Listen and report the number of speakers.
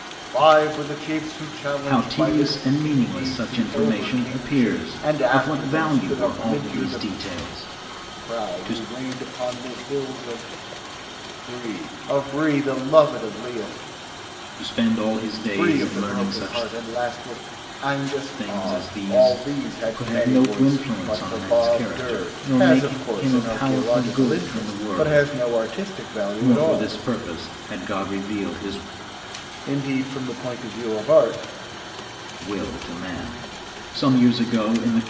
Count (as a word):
two